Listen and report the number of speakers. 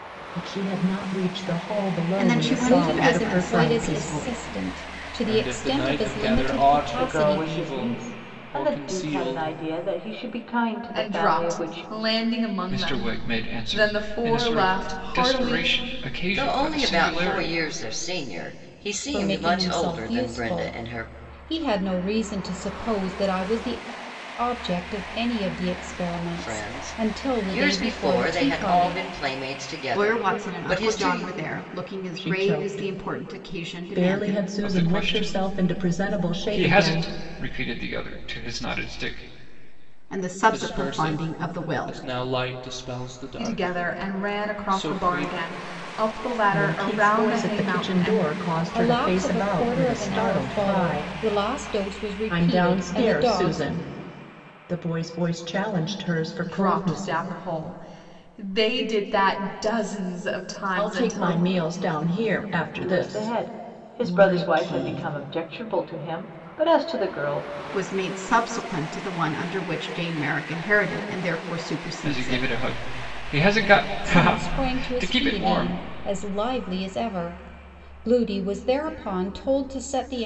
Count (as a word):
eight